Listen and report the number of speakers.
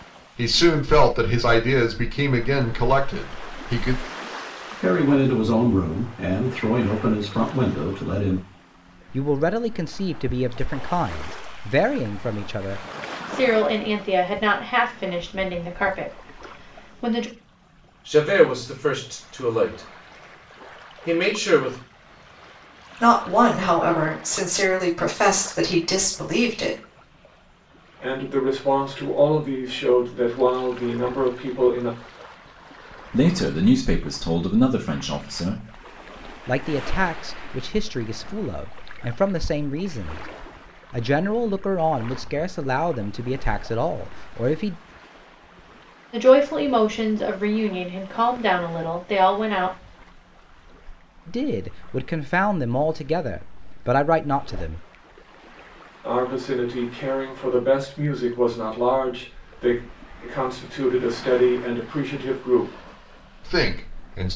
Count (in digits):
8